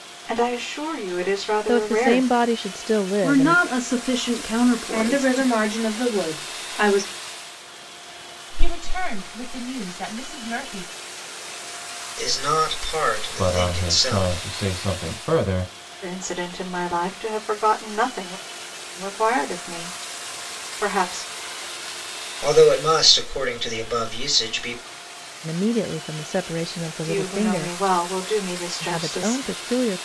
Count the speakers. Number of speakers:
7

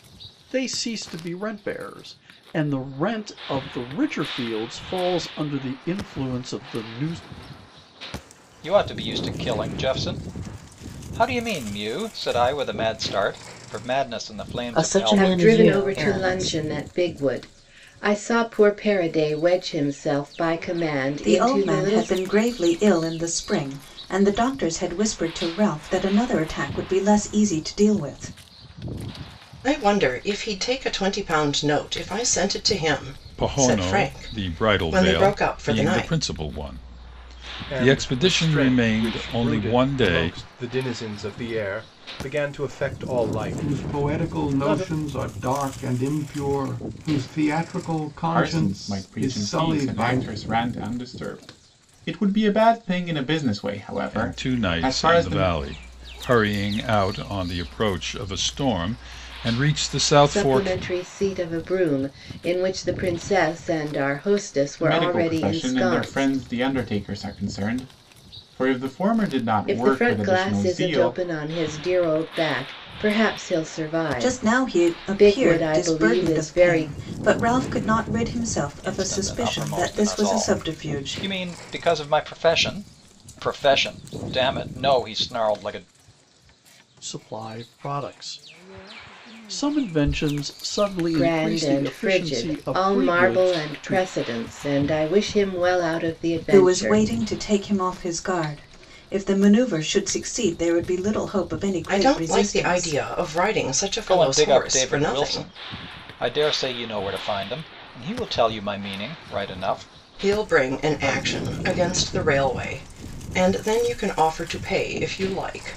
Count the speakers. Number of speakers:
10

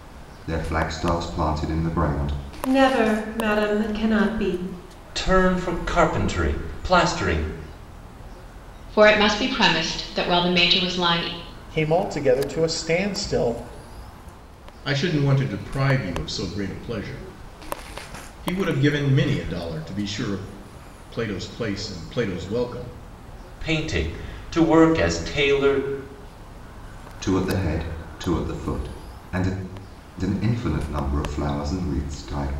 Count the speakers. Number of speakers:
6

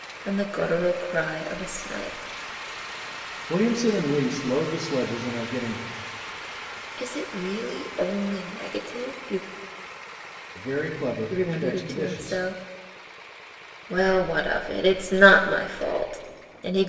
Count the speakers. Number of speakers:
2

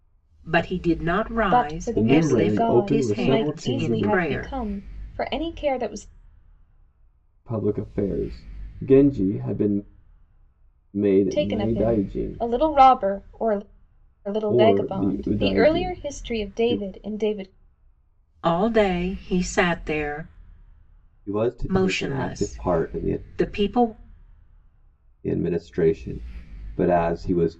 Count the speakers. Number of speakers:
3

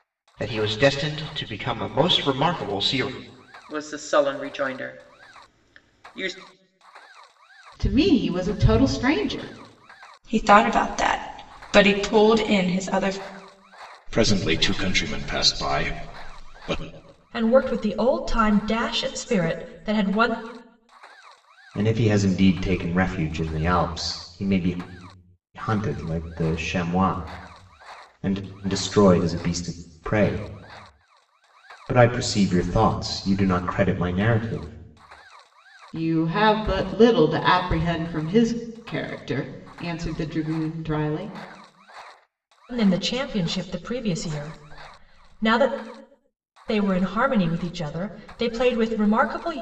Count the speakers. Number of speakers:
7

